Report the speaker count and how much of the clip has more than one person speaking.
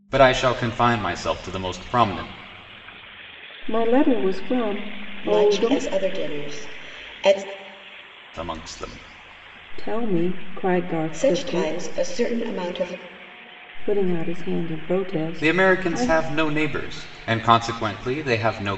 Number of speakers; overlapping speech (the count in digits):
3, about 11%